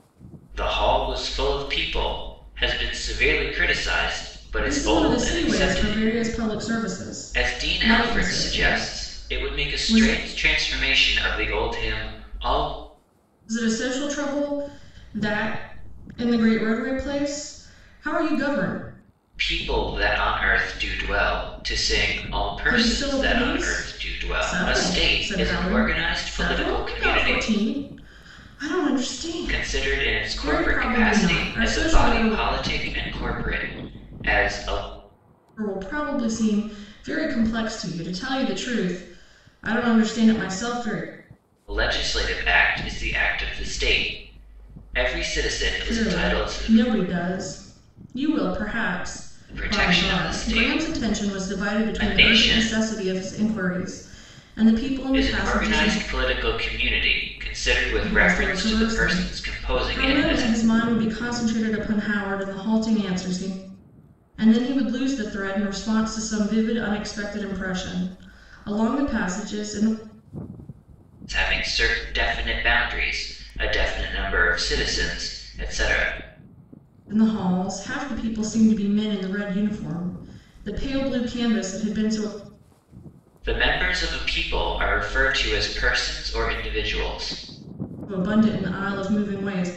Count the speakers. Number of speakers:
two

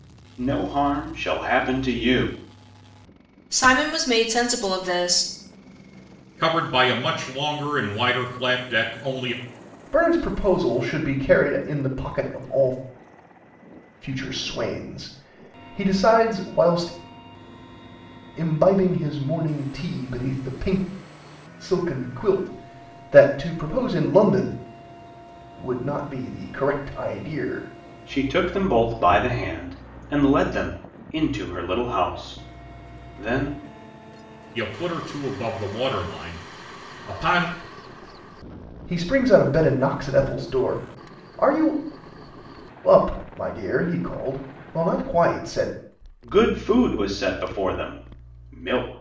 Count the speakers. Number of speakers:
four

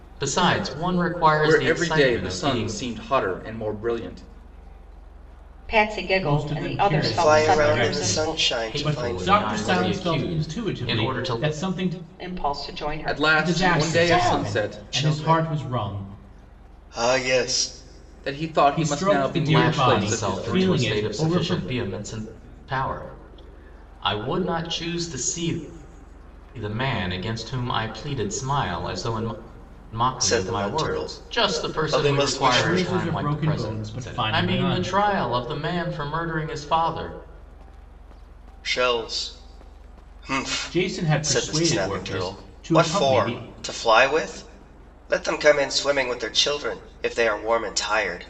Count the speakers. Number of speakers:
five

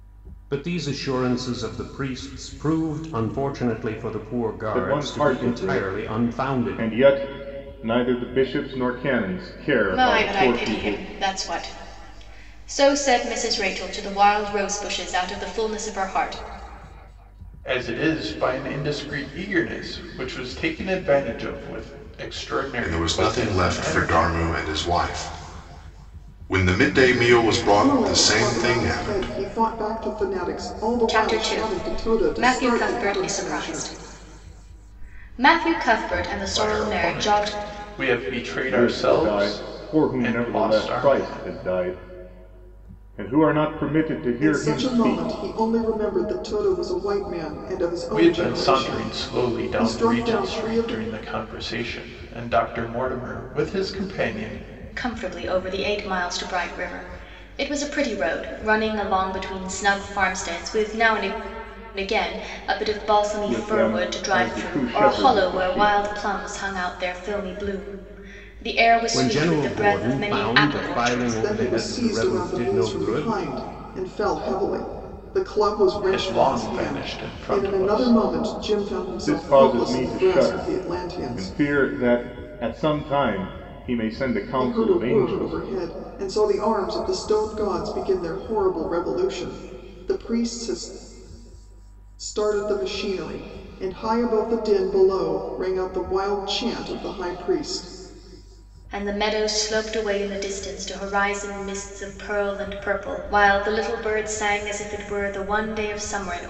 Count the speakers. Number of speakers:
six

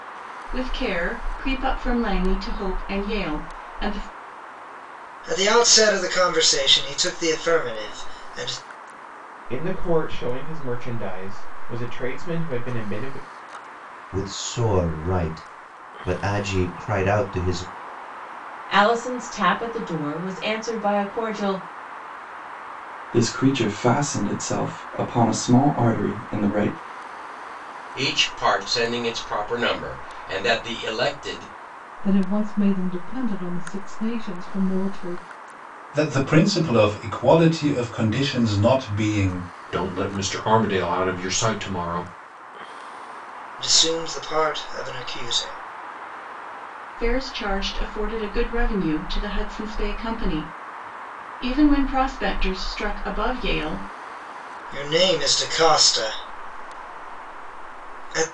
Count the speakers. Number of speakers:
ten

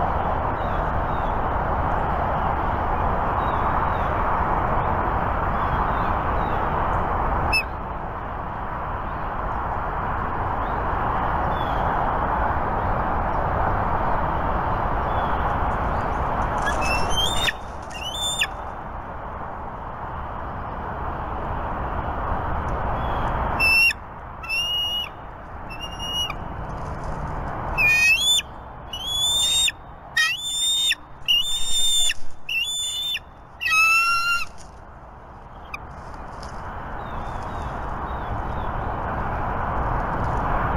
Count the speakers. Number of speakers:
zero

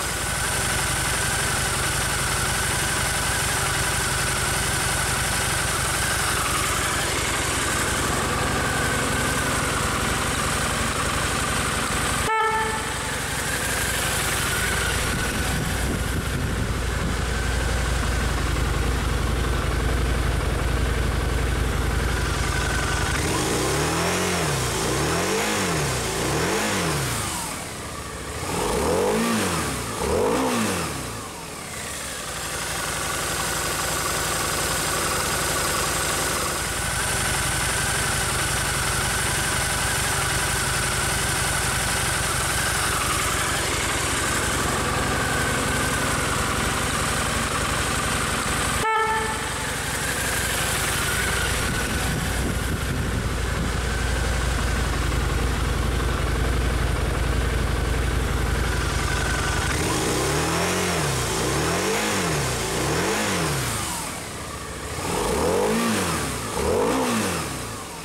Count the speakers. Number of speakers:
zero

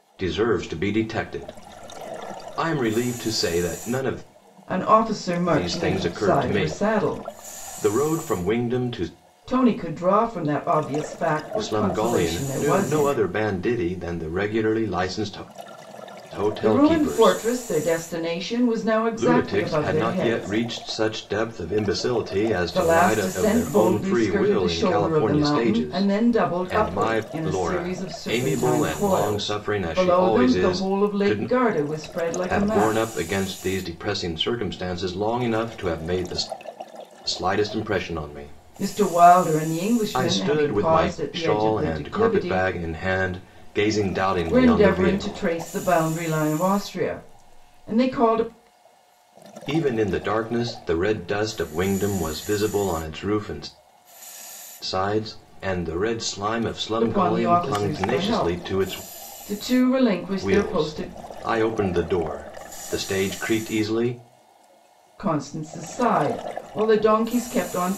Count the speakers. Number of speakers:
two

